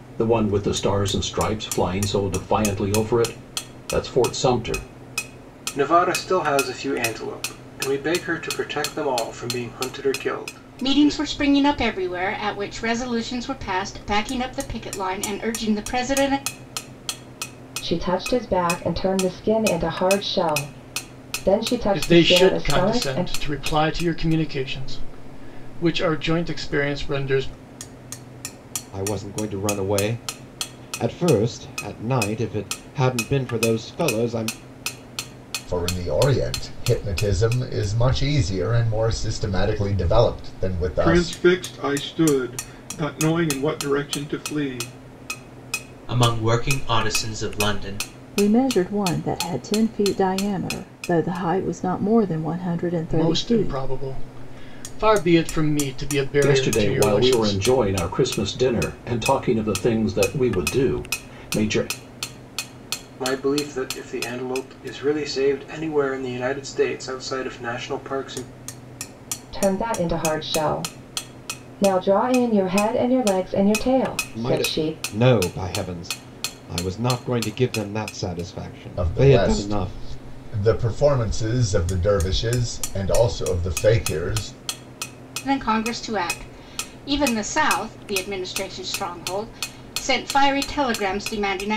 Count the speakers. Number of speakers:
10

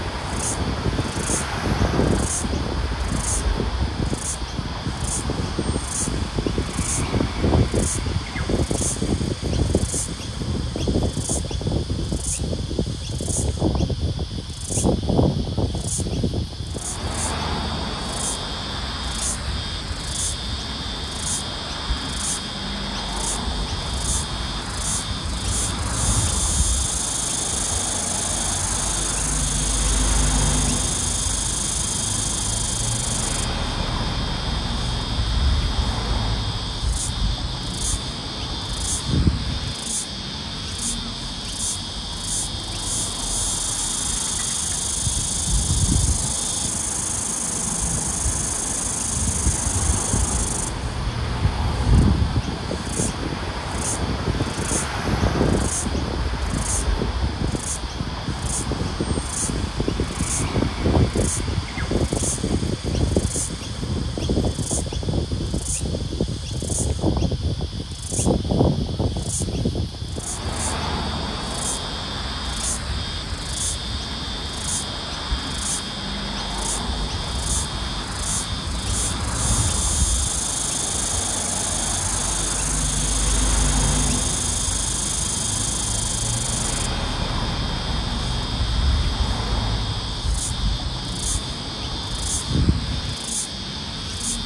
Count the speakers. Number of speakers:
0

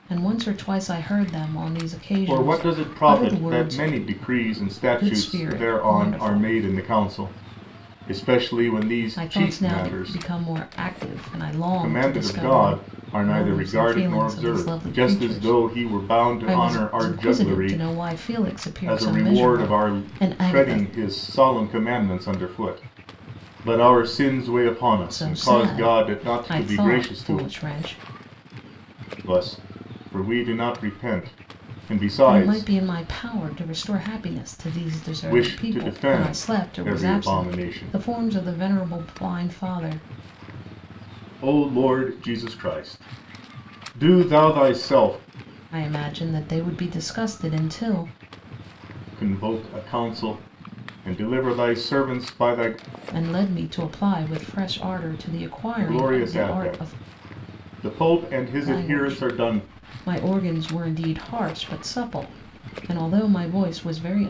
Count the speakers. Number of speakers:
2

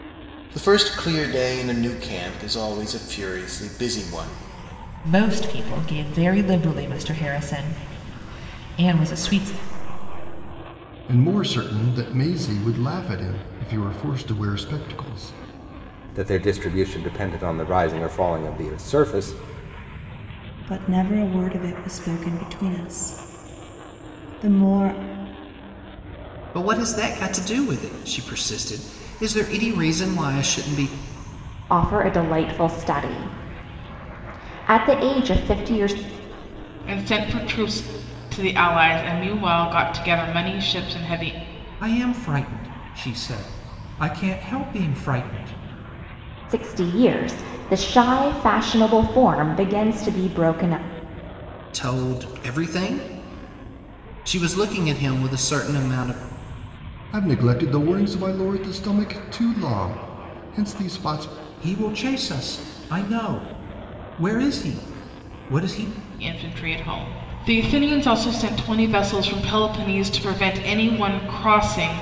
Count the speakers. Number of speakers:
9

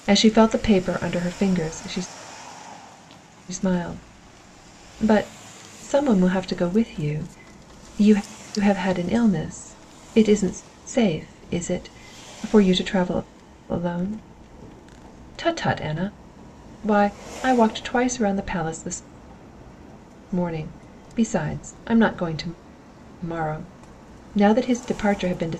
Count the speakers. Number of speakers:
1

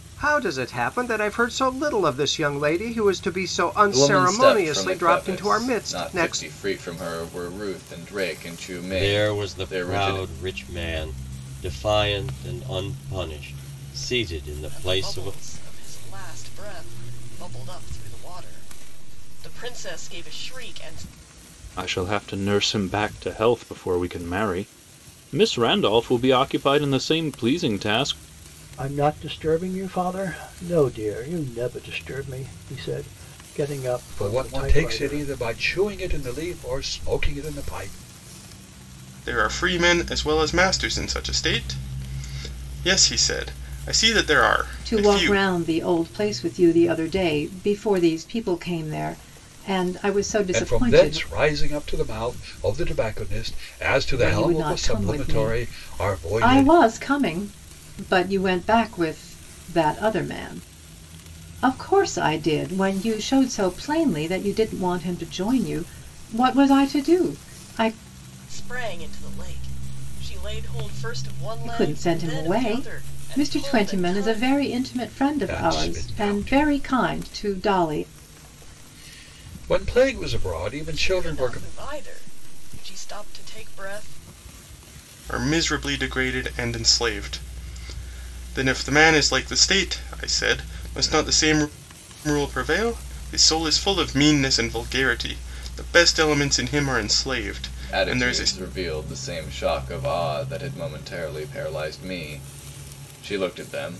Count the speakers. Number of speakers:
9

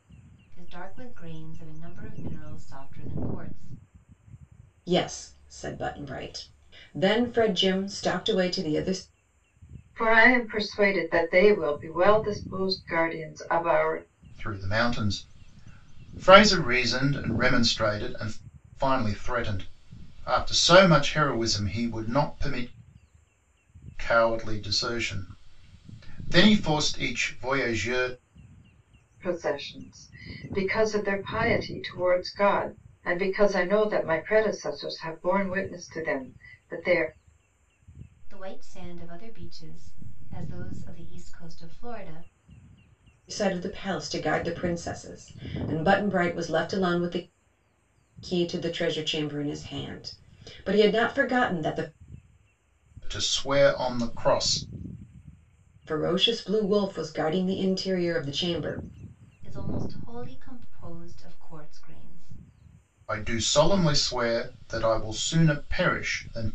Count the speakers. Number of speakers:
4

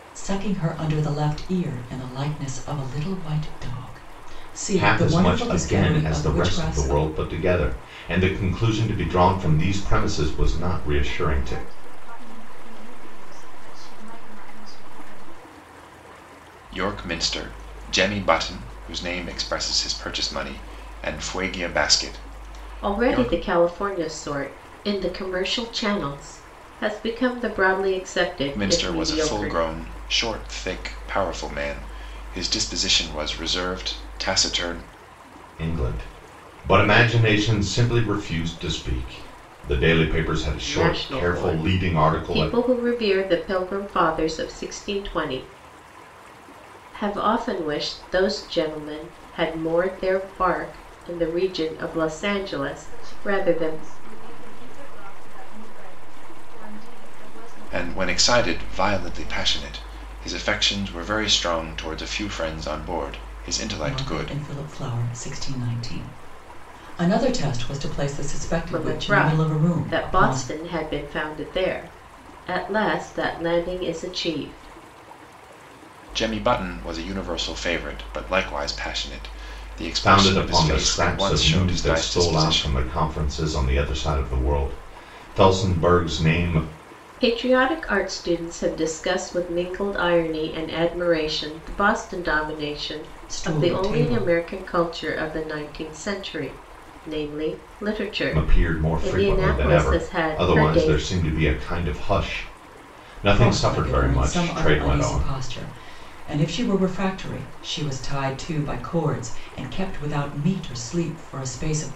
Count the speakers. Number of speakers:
5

